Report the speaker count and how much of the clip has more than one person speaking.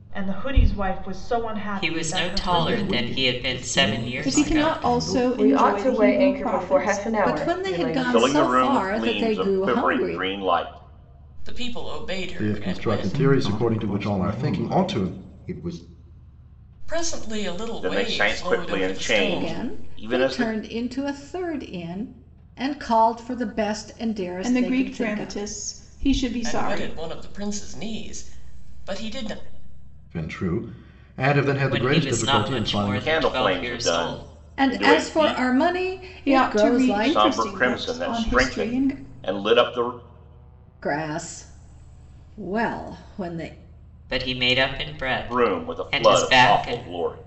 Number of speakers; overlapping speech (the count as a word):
nine, about 50%